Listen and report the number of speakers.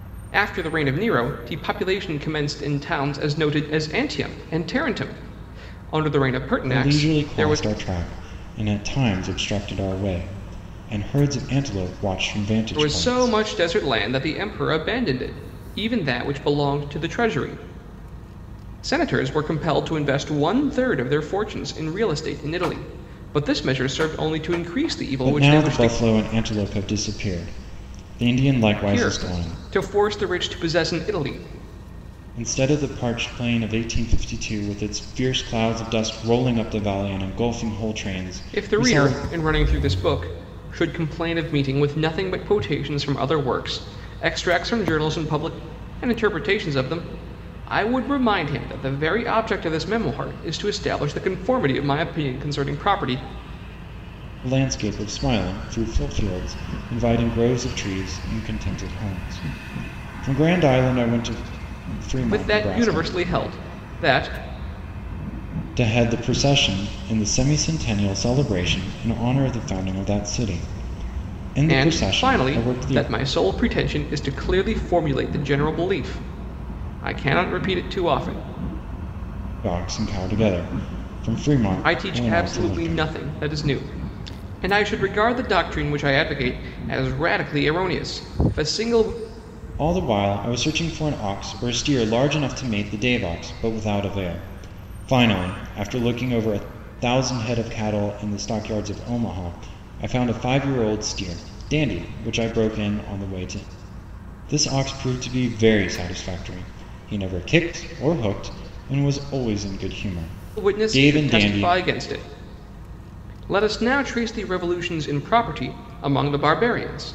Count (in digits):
2